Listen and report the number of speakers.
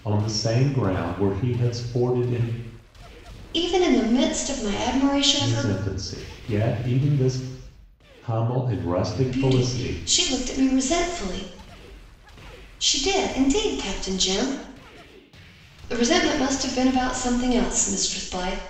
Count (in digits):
2